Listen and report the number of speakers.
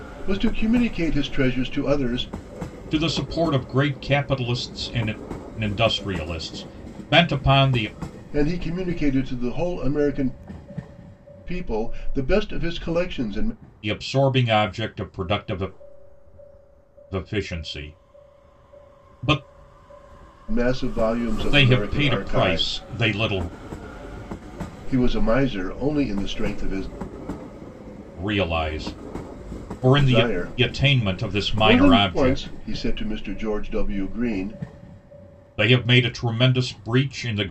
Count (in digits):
2